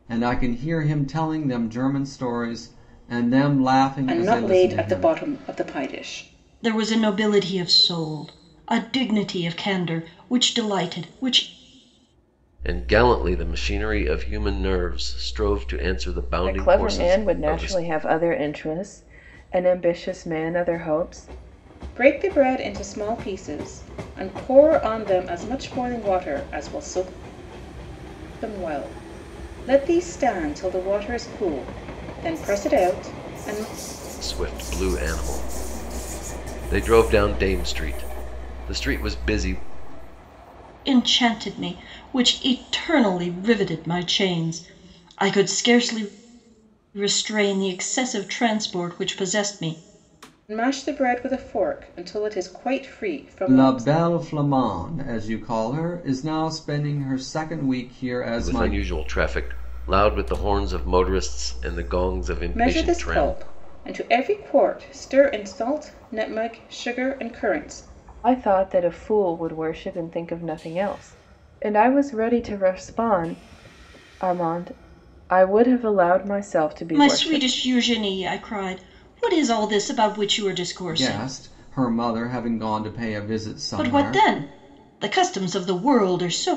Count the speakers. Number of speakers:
five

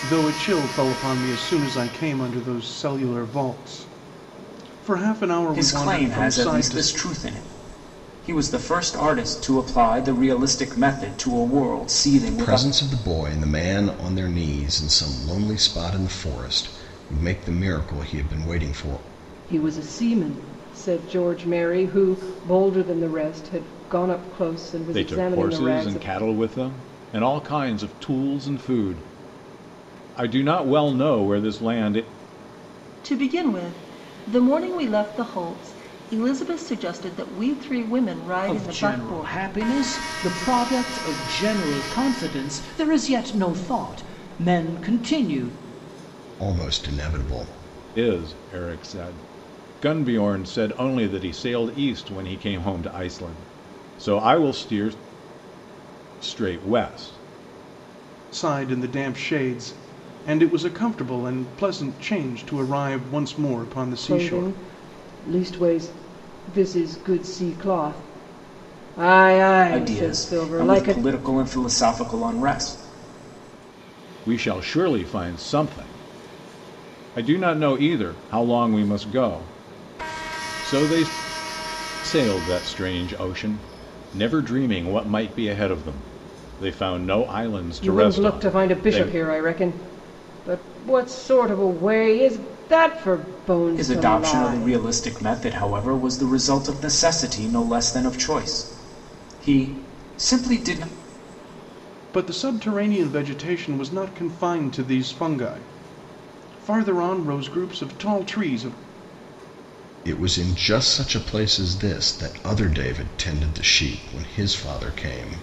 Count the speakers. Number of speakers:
seven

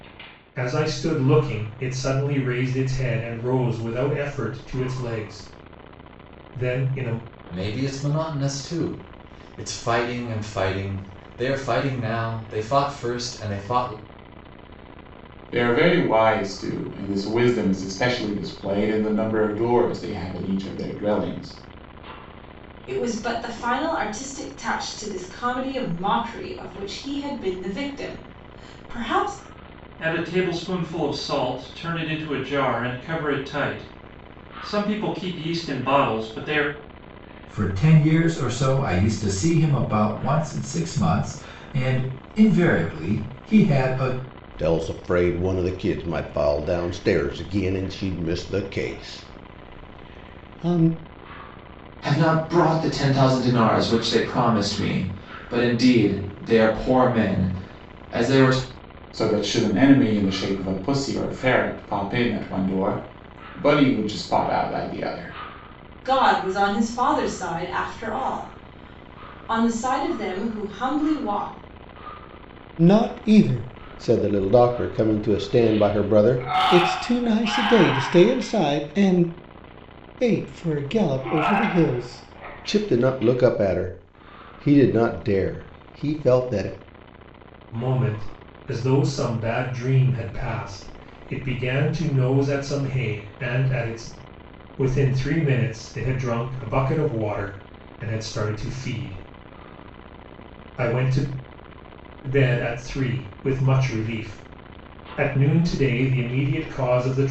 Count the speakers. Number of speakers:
eight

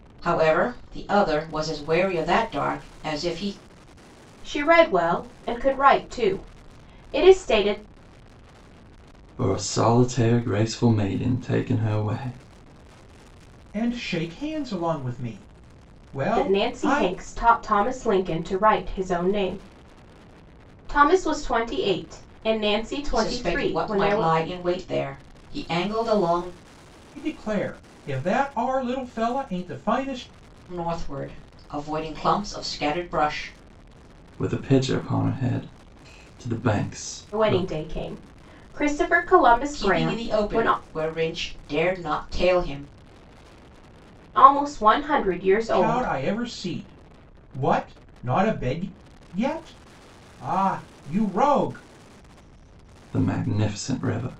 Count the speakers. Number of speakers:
four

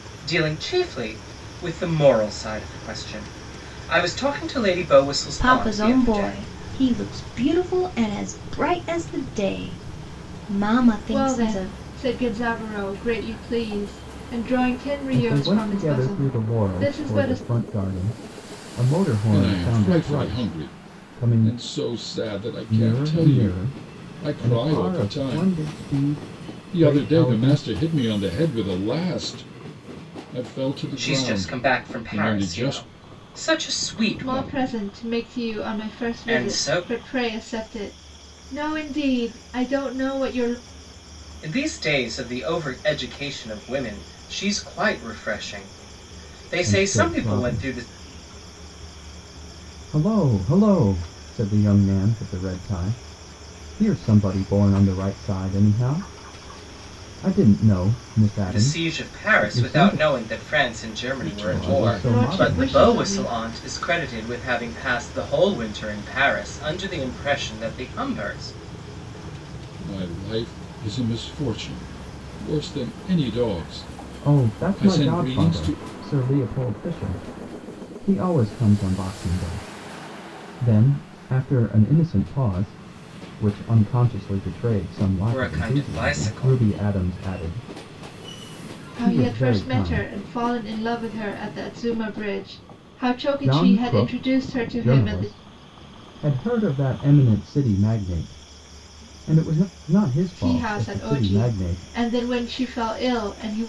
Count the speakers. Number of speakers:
five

